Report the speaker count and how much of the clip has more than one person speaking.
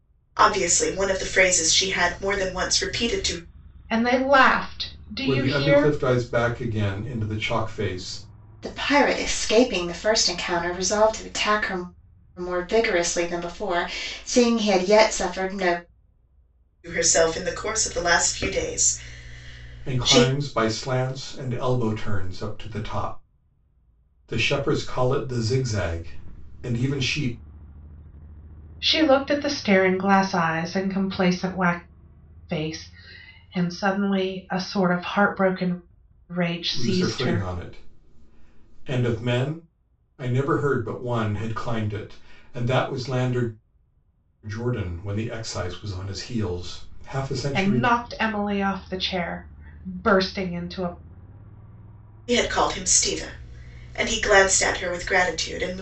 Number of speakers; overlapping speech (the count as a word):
four, about 4%